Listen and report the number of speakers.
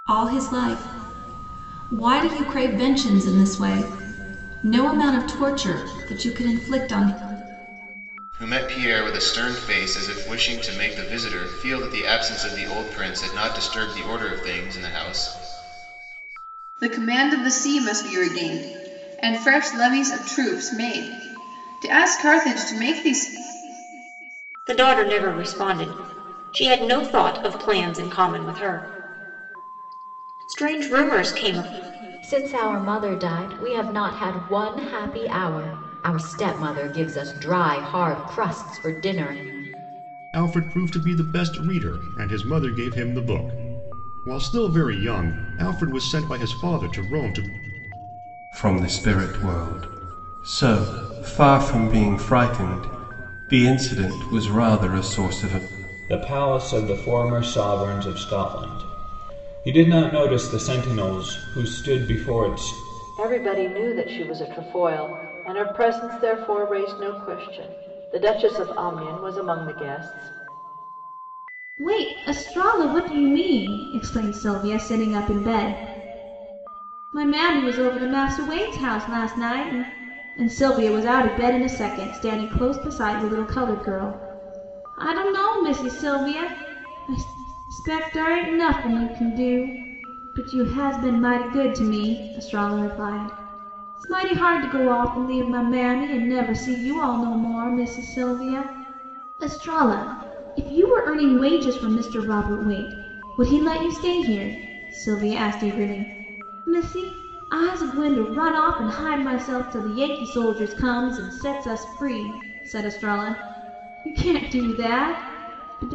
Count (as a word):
ten